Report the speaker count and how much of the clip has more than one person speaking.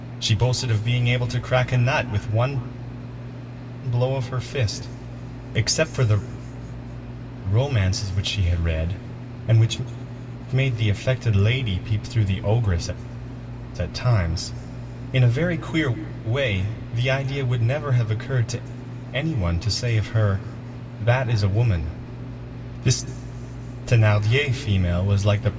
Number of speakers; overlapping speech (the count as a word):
one, no overlap